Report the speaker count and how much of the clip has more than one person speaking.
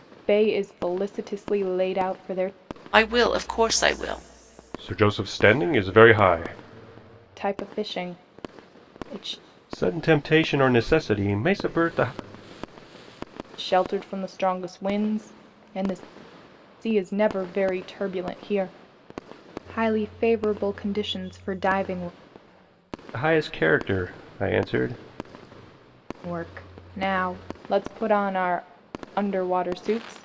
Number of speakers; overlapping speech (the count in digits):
3, no overlap